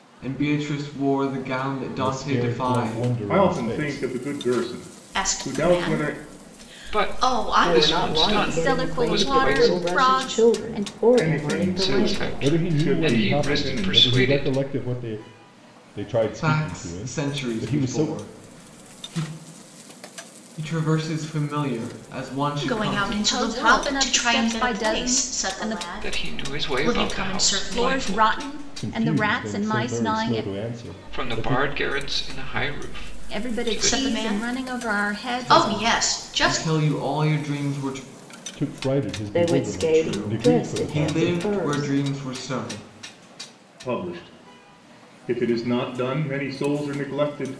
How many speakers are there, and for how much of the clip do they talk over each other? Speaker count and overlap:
7, about 56%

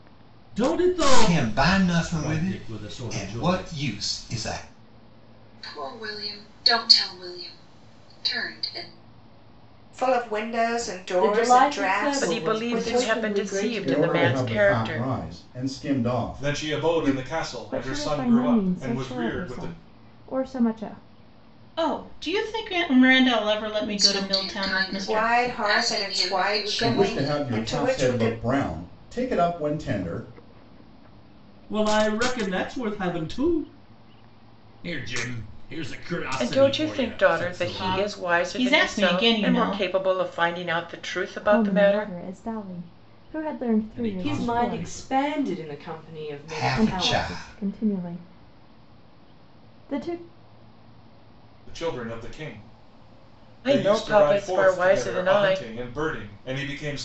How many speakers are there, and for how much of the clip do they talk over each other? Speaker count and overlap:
10, about 40%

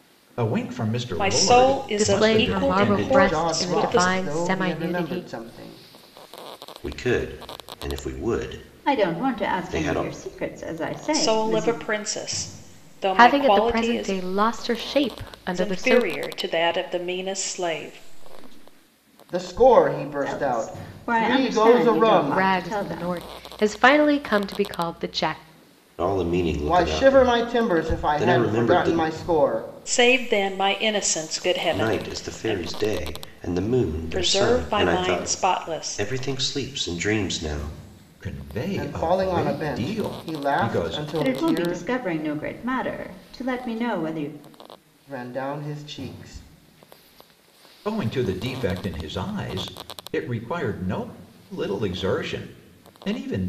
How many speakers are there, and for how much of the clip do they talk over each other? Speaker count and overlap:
6, about 36%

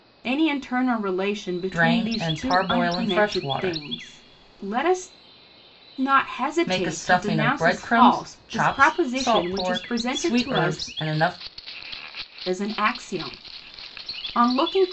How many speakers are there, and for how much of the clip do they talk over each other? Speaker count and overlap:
2, about 41%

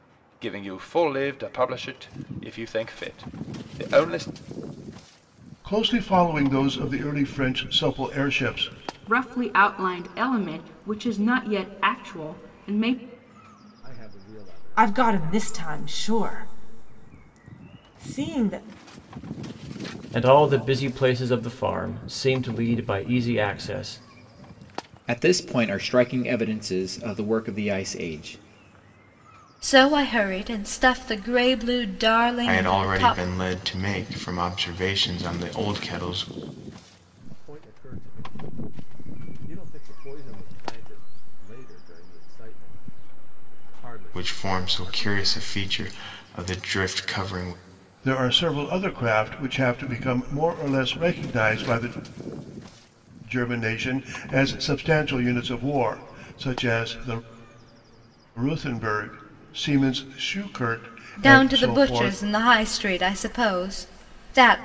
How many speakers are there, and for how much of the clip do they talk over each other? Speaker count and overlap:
9, about 7%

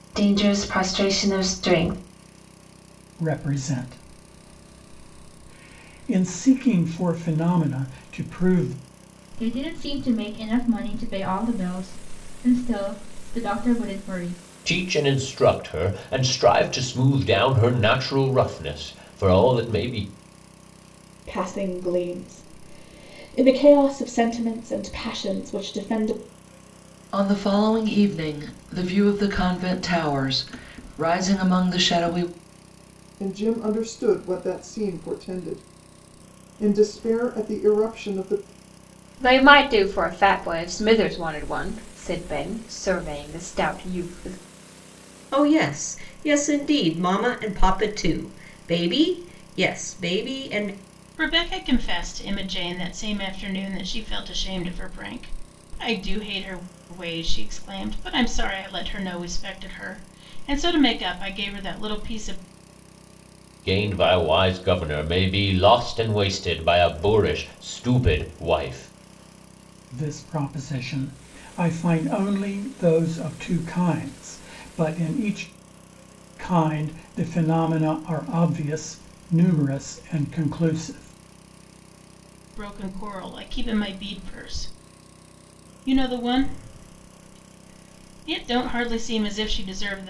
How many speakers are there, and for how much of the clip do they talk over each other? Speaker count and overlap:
10, no overlap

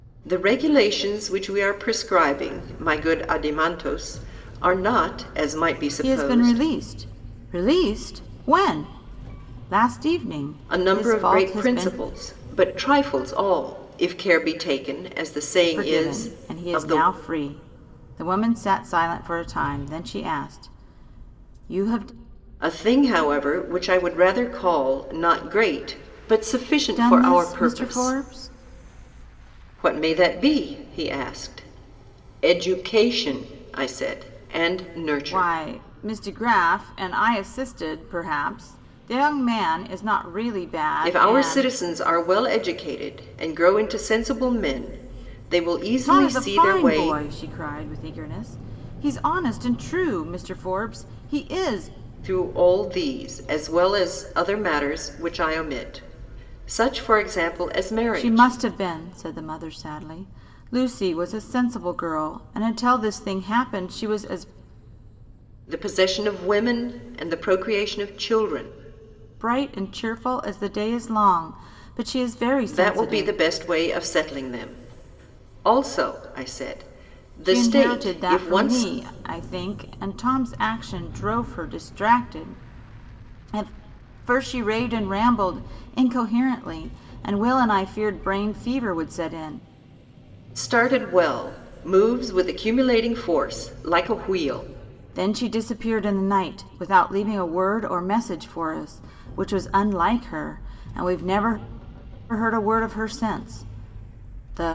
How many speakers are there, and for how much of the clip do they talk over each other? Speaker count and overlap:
2, about 9%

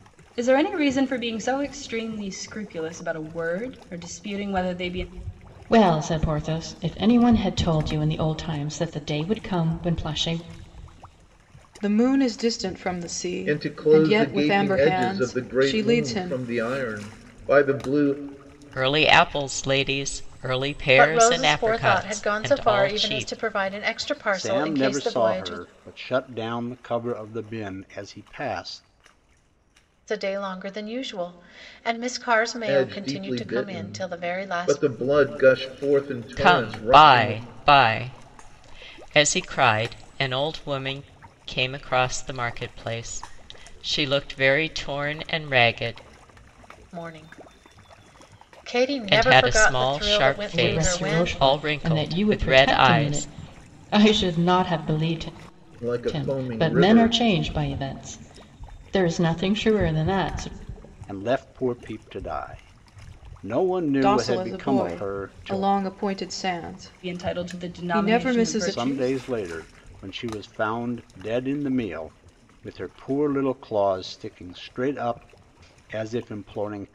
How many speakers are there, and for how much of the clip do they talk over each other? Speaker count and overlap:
7, about 25%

